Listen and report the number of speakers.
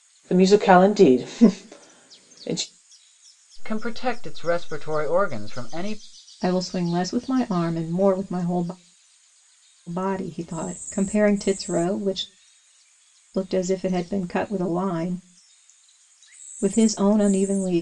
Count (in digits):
3